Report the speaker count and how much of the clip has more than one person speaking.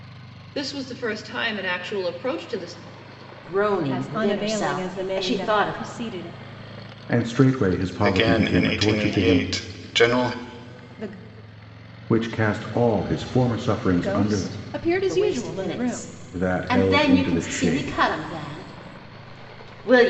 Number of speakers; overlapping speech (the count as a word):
five, about 39%